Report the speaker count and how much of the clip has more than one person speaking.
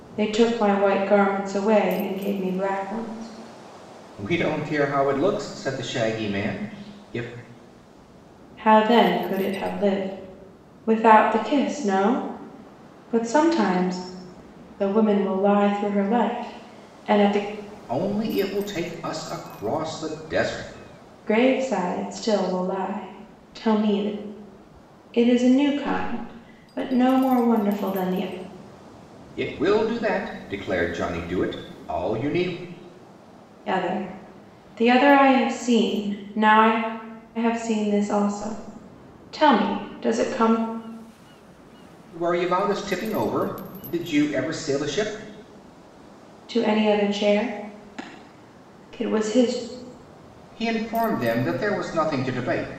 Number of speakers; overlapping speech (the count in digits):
2, no overlap